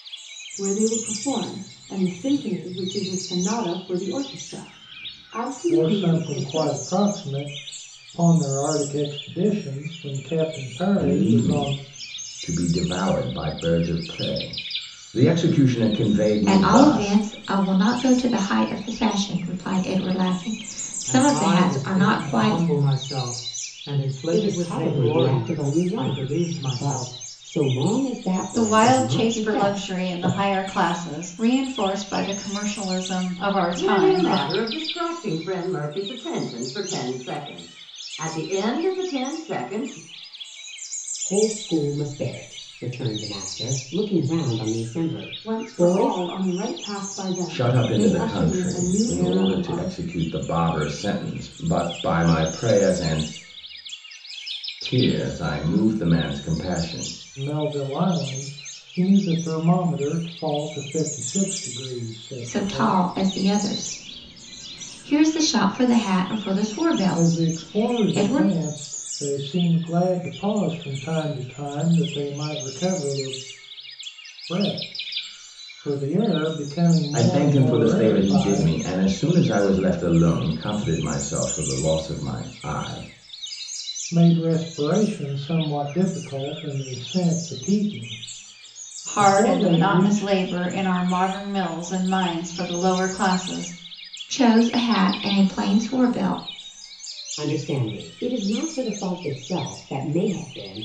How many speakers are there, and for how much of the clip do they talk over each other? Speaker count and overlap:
8, about 18%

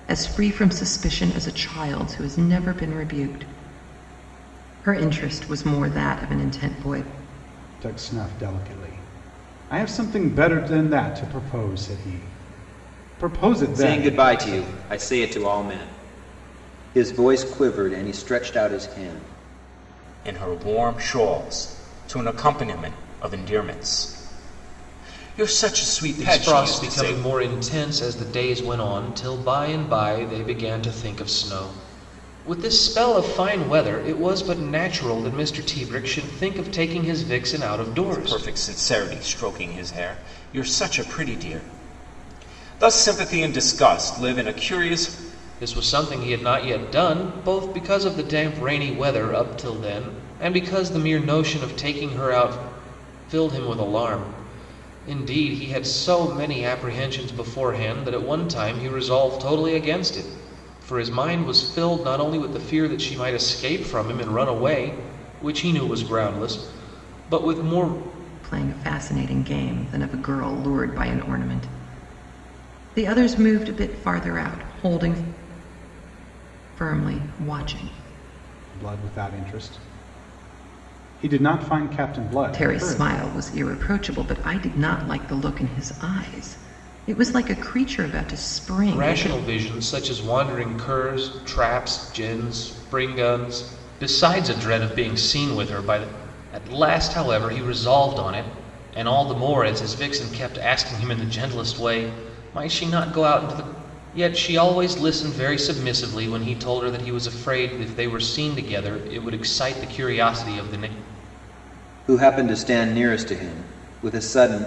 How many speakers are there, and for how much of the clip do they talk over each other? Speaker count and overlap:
5, about 3%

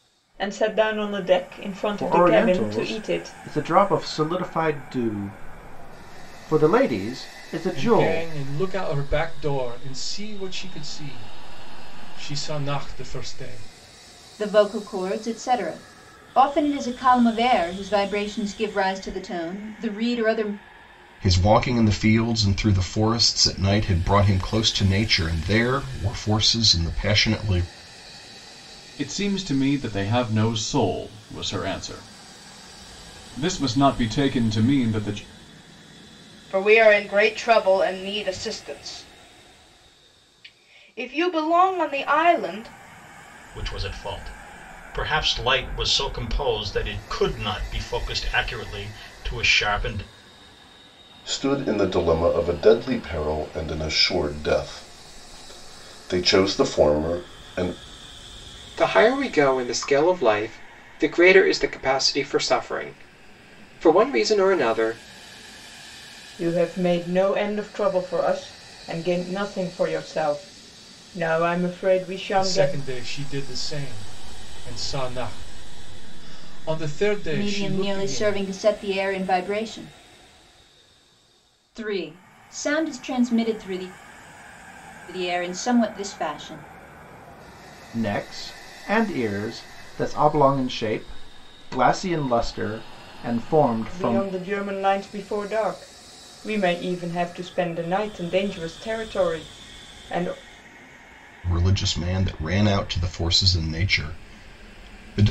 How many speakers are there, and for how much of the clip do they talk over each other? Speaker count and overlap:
10, about 4%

